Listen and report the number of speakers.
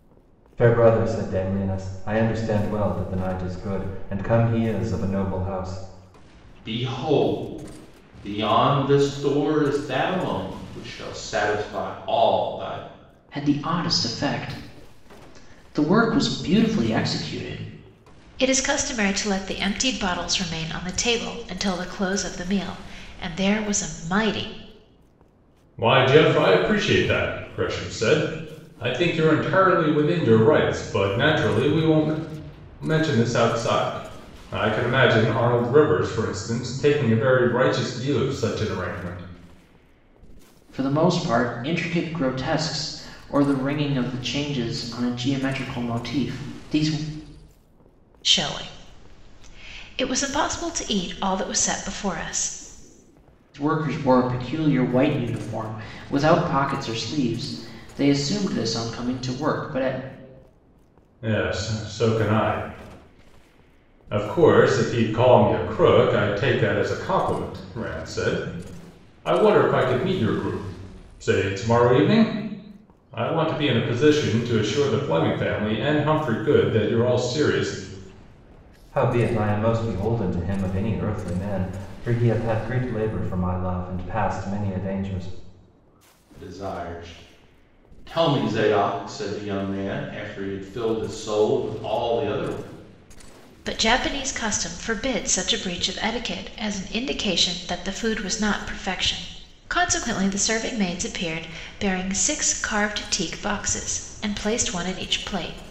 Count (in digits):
5